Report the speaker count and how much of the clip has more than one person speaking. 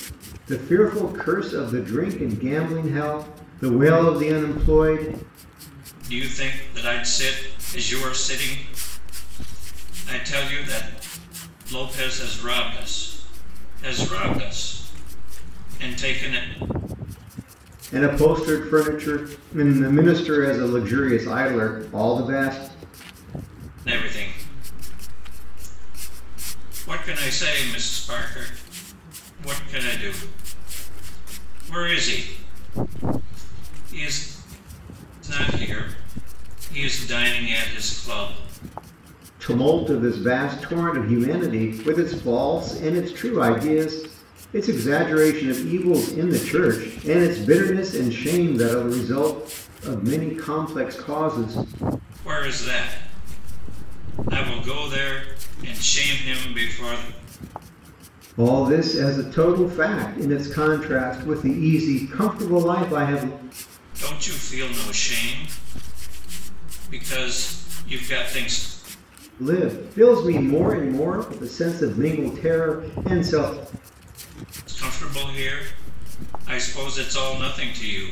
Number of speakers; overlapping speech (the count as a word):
two, no overlap